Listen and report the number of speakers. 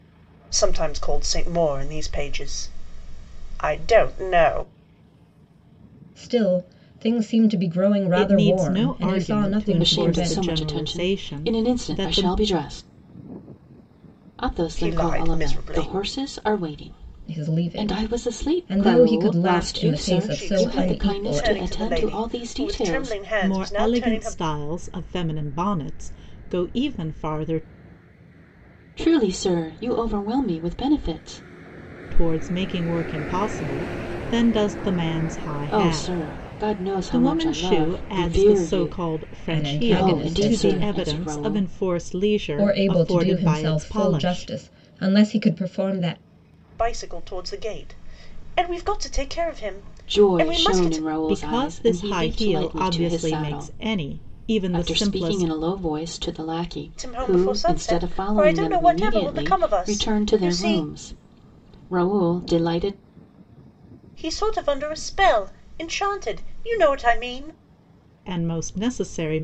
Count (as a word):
four